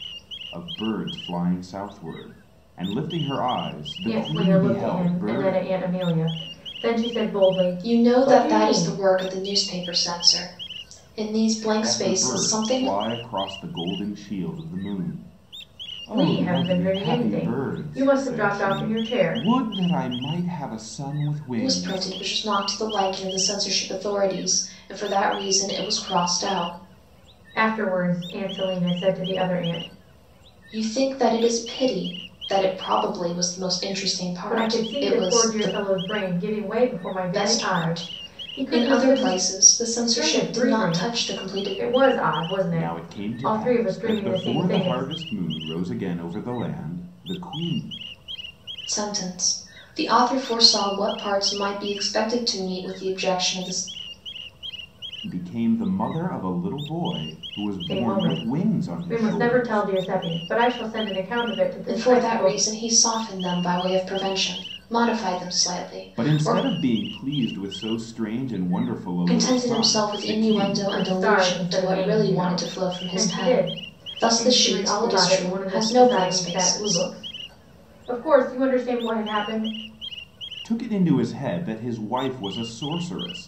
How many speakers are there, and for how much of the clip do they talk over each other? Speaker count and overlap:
3, about 31%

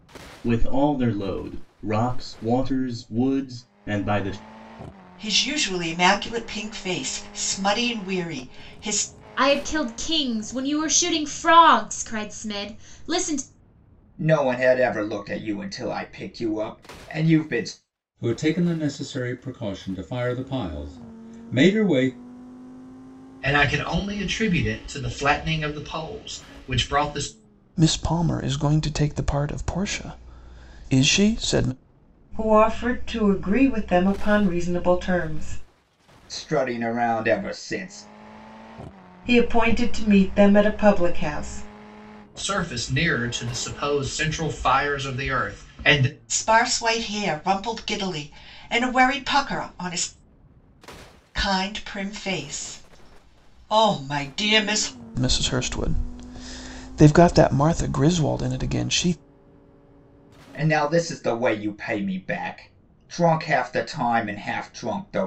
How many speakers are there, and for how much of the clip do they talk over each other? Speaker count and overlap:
8, no overlap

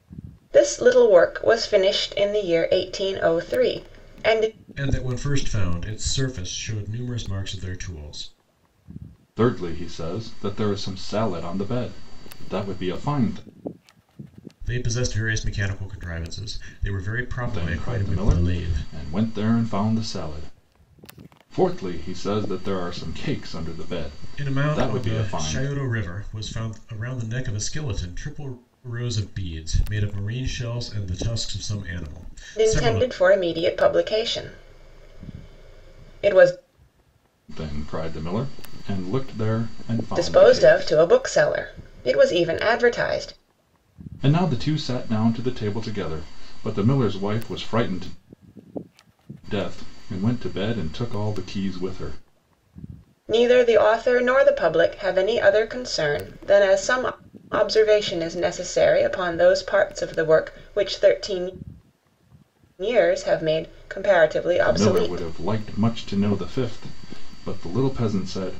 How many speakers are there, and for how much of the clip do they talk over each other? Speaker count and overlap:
3, about 7%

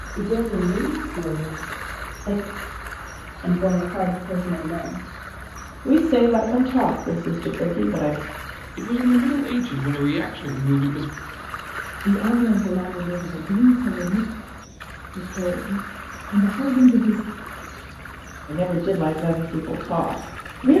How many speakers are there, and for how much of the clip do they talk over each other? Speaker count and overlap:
5, no overlap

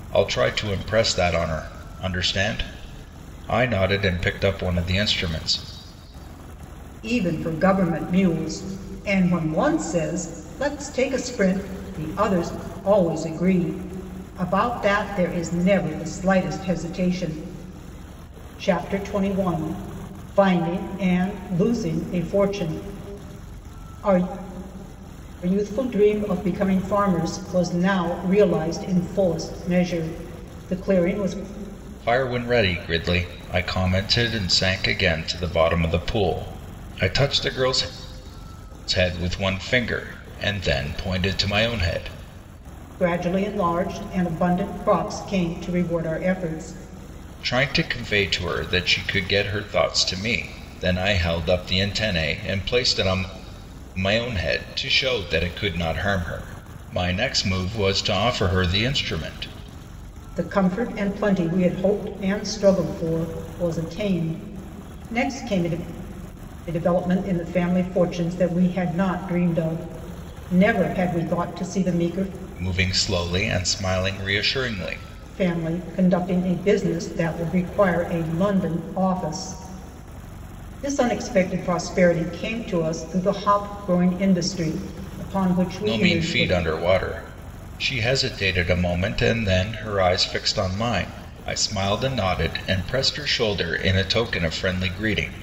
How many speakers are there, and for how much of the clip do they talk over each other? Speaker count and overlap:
2, about 1%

